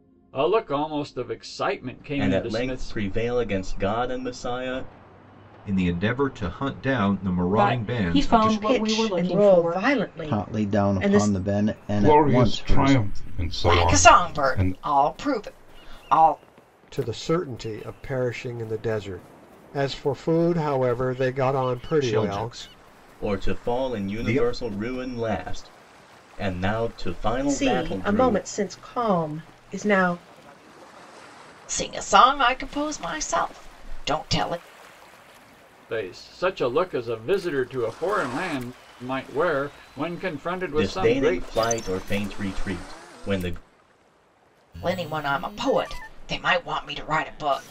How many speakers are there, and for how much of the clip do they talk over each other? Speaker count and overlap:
9, about 21%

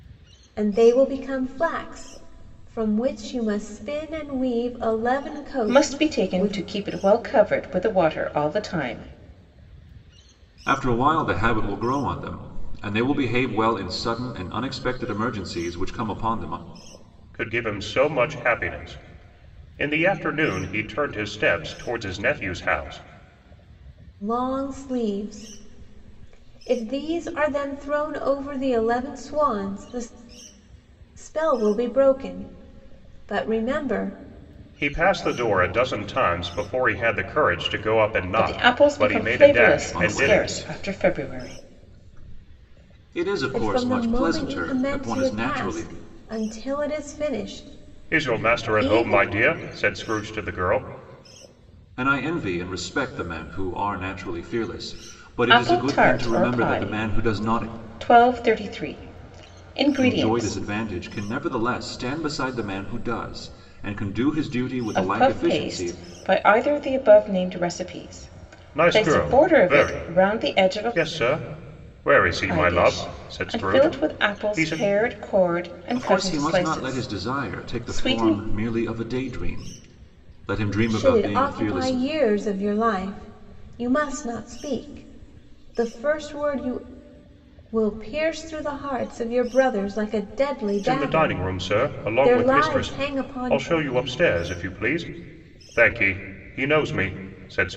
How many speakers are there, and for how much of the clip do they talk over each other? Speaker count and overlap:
4, about 24%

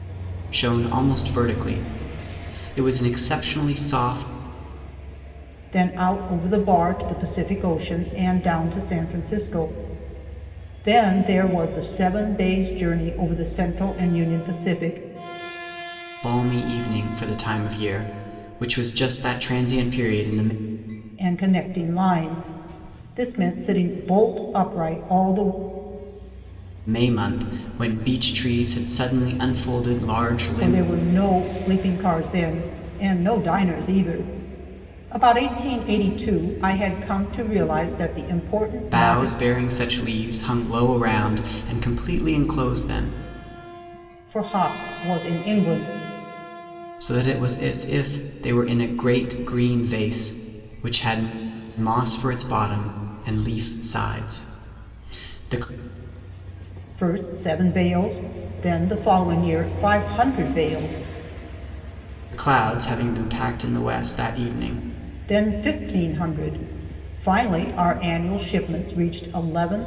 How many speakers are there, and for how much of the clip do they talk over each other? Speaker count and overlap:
2, about 1%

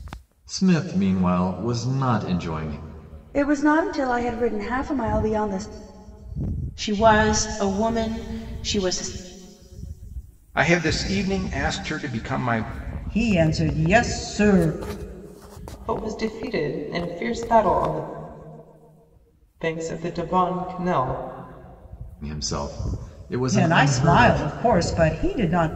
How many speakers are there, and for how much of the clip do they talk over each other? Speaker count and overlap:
6, about 4%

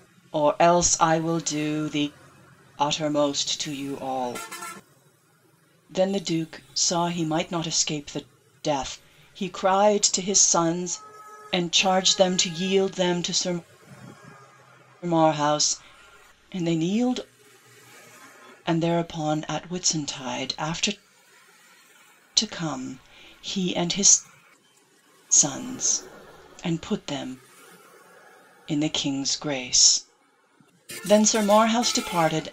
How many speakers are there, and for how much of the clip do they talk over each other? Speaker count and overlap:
1, no overlap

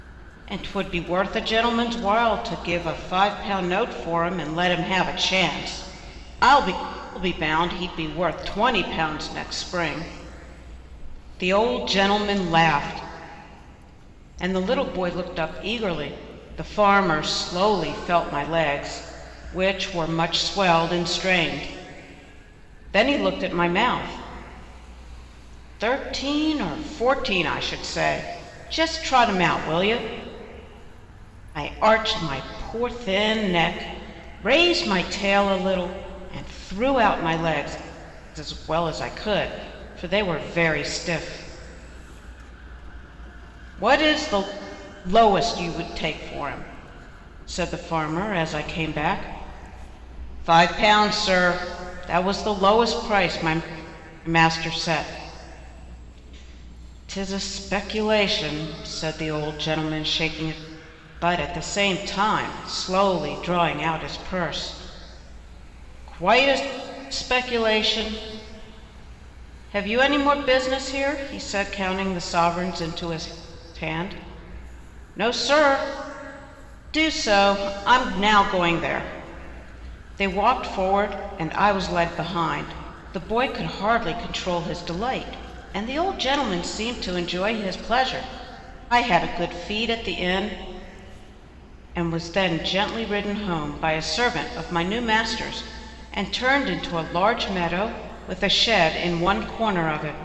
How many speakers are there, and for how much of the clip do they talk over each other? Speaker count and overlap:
1, no overlap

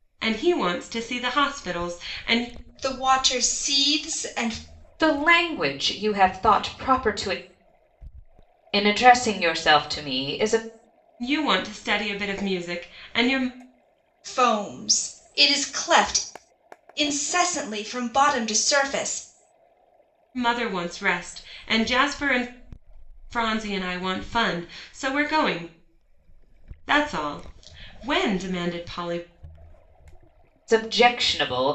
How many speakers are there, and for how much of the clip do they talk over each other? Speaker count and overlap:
3, no overlap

